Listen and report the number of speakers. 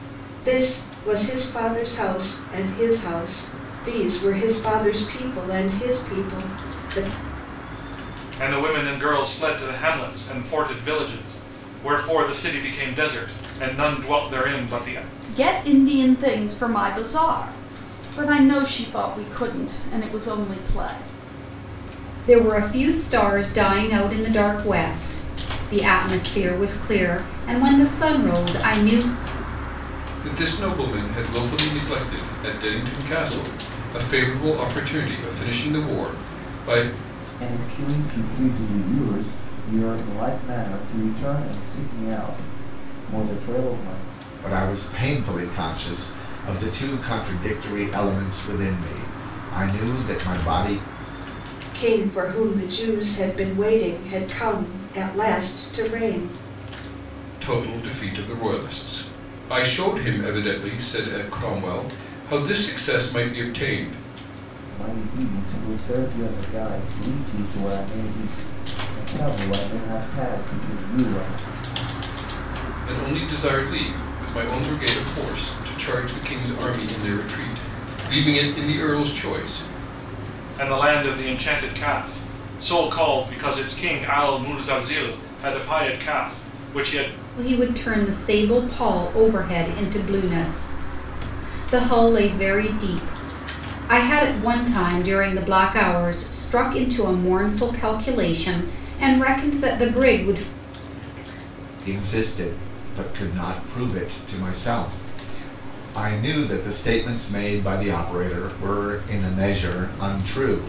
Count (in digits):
7